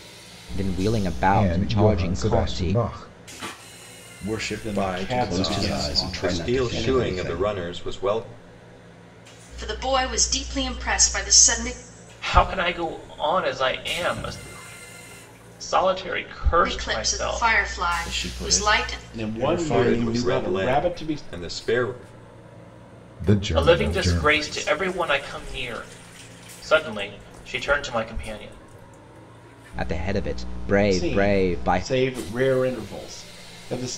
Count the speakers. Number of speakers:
8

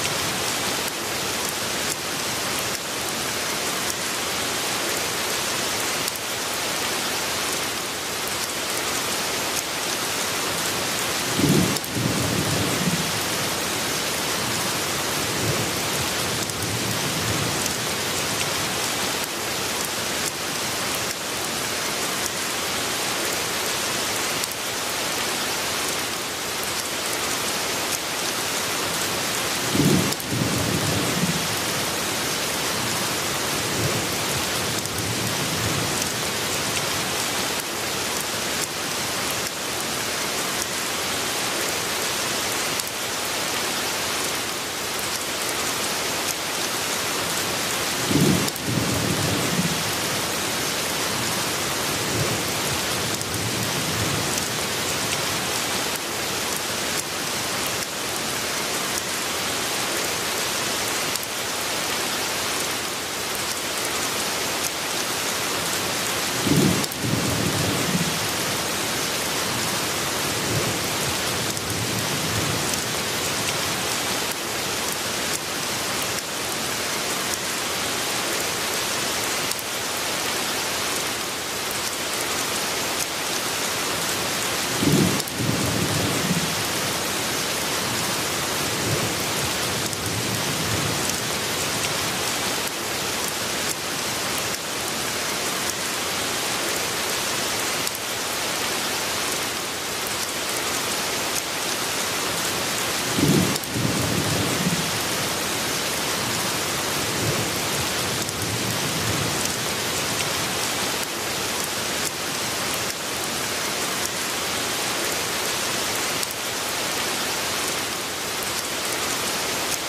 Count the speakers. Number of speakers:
0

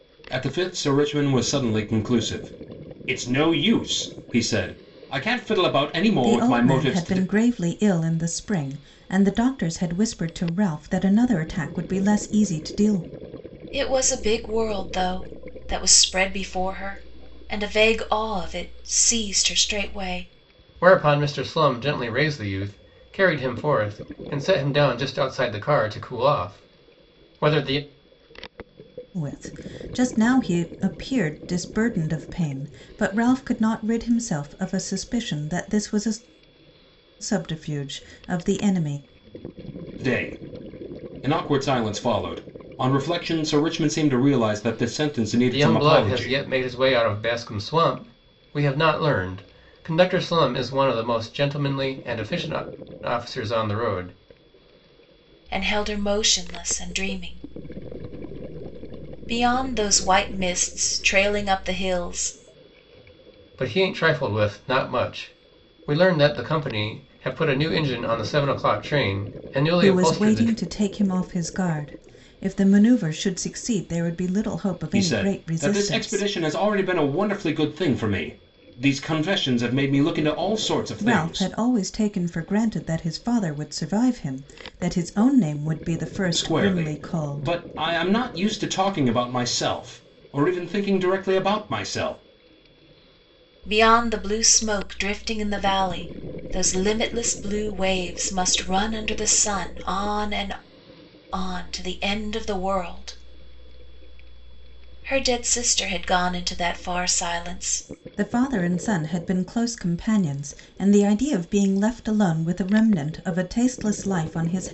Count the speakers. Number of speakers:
4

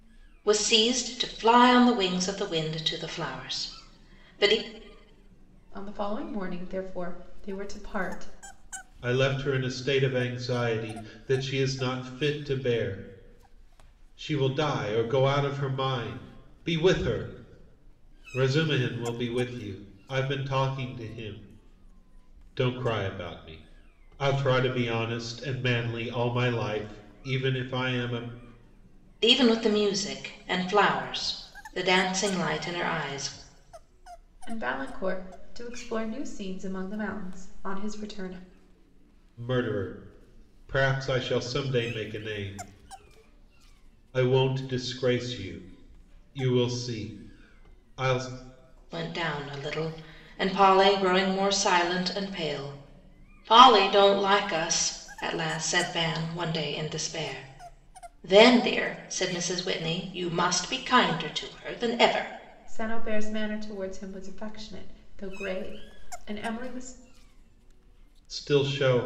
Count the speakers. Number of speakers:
3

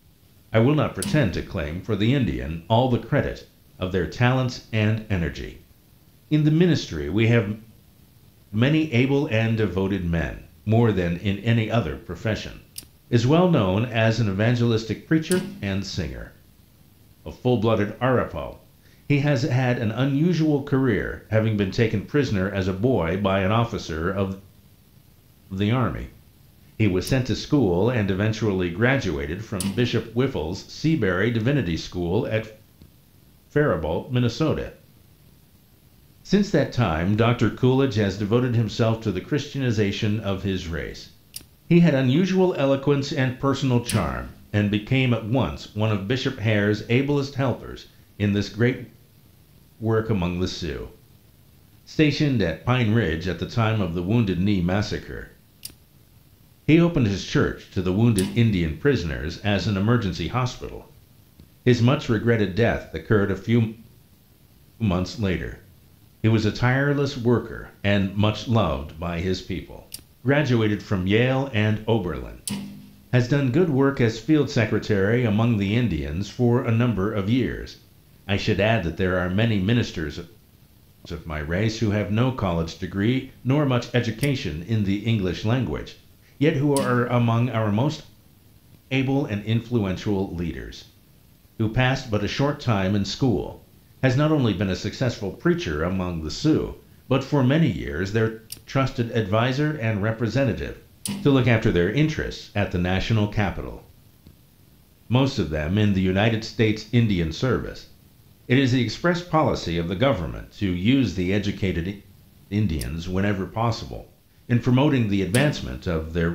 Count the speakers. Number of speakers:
1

